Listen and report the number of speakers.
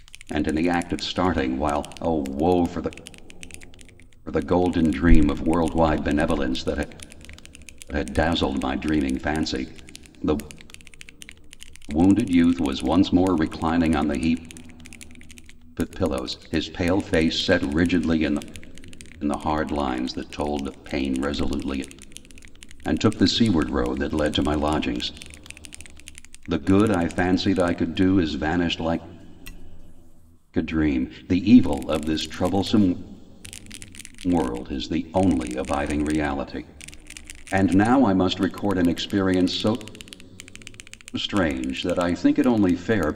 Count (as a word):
one